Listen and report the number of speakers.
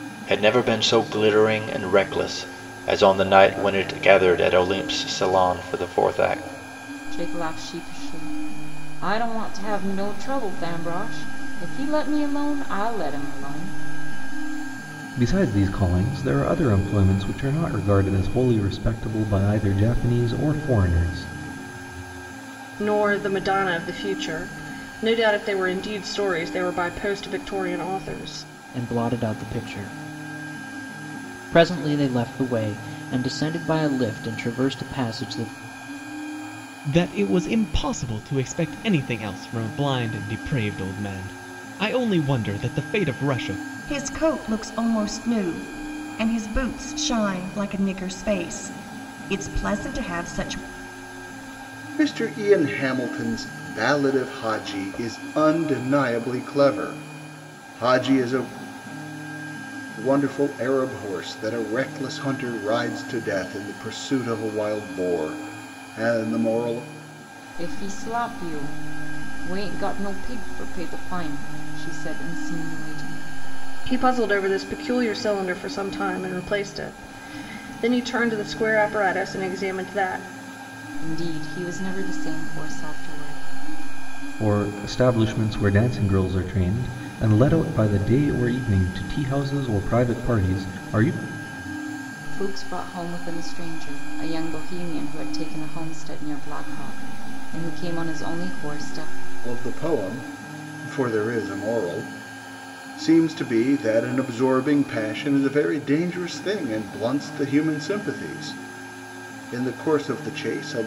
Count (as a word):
eight